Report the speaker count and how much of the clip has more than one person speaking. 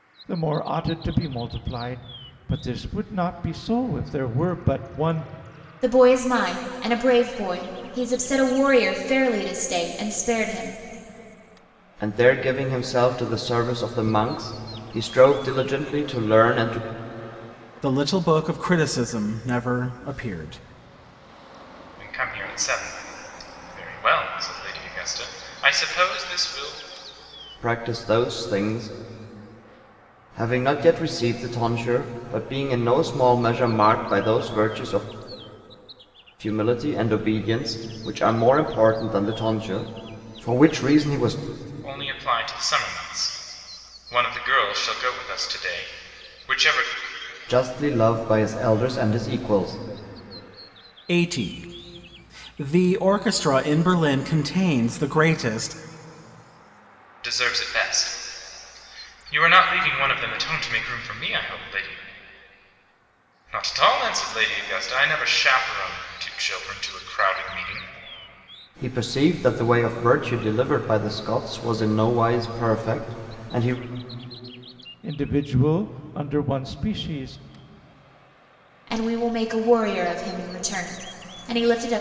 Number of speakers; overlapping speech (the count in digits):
5, no overlap